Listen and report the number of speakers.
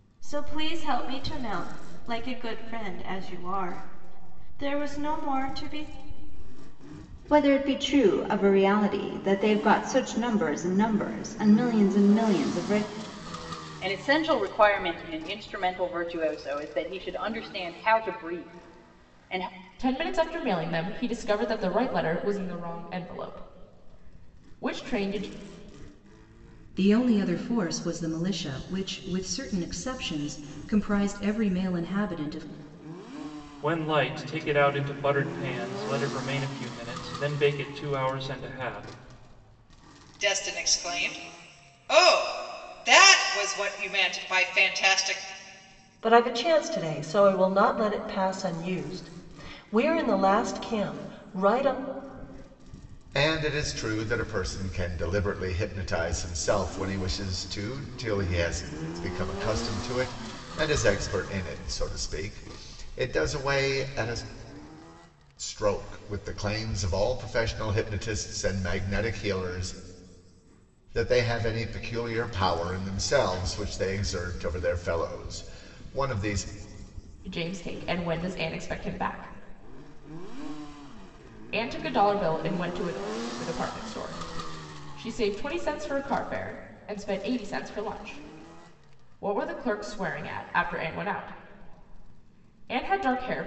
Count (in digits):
9